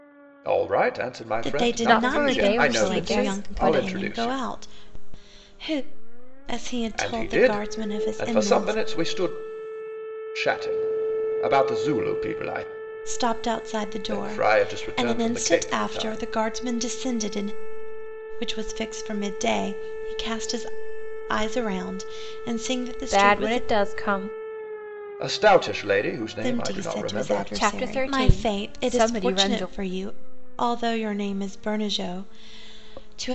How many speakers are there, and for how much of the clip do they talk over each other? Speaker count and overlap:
3, about 34%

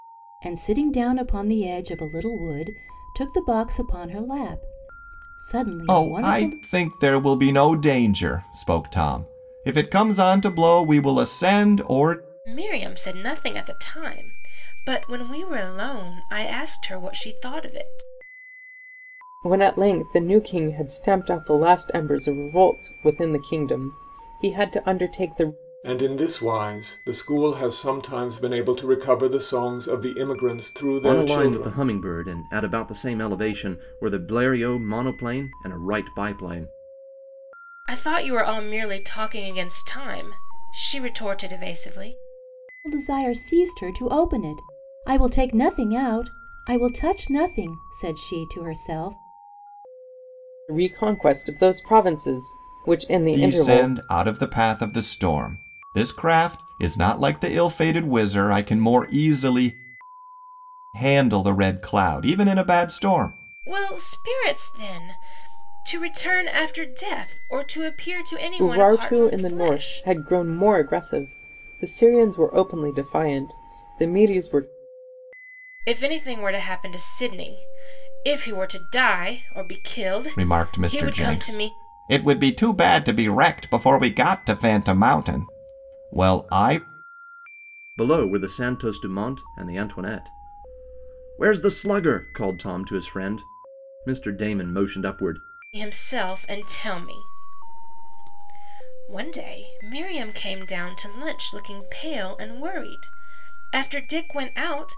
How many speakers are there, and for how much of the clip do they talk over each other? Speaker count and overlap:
6, about 5%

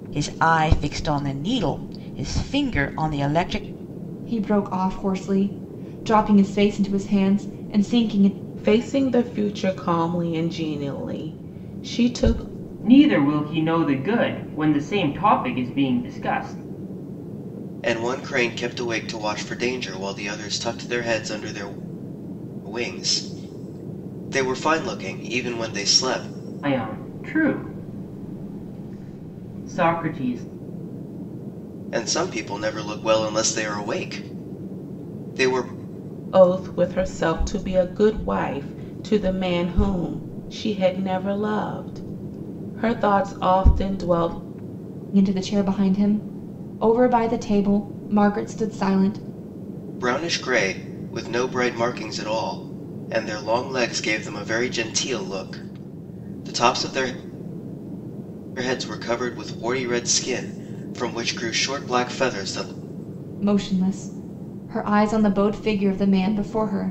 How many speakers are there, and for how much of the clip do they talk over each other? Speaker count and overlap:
5, no overlap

